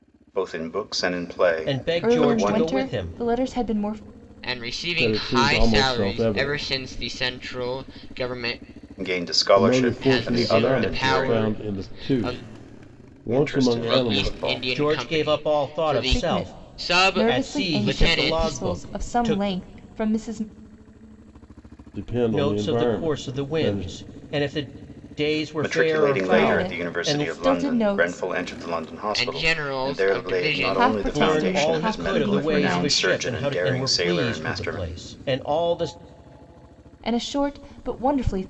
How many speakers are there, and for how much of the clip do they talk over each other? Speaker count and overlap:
5, about 58%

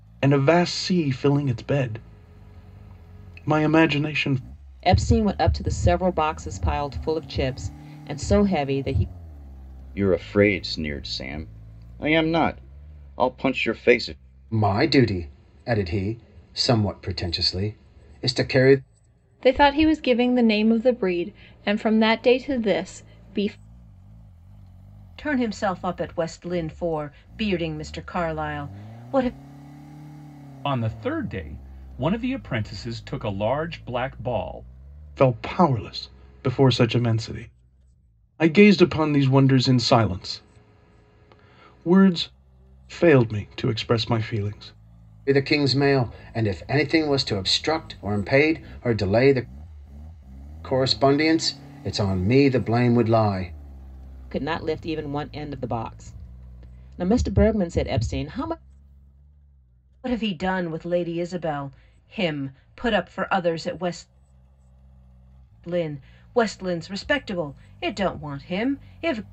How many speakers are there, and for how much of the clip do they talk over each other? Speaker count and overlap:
7, no overlap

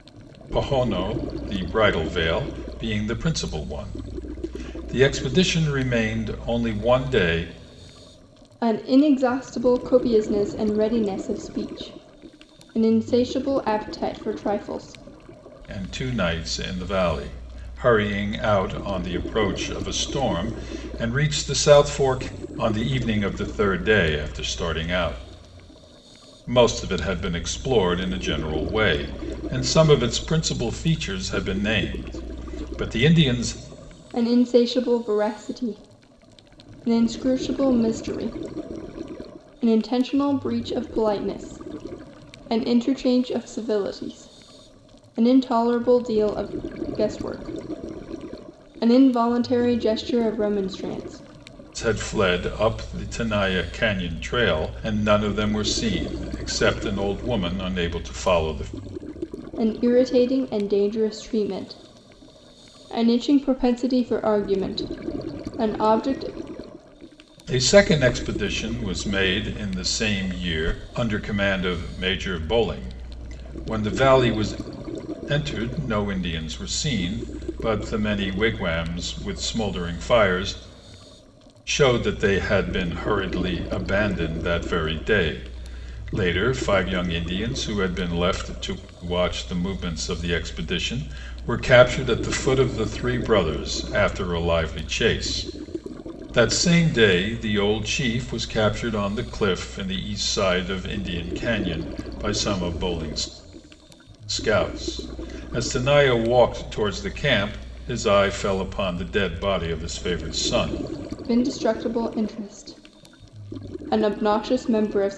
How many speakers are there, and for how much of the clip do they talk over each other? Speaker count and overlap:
2, no overlap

